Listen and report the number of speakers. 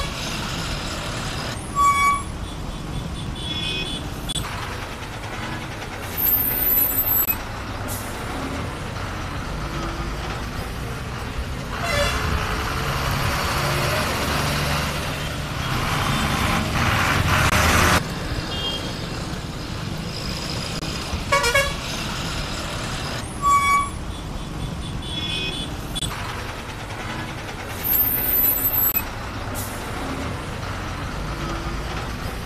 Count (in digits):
0